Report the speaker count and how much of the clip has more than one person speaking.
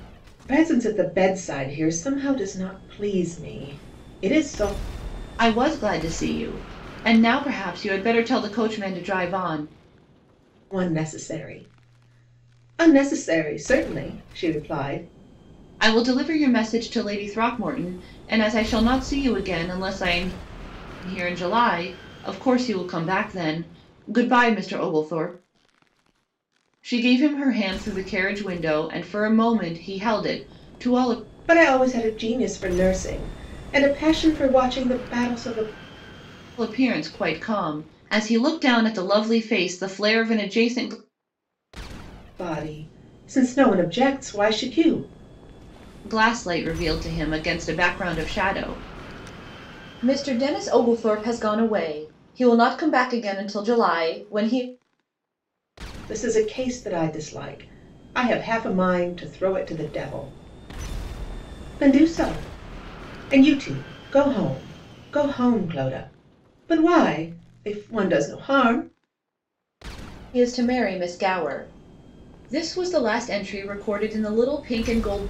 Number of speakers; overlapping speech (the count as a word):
two, no overlap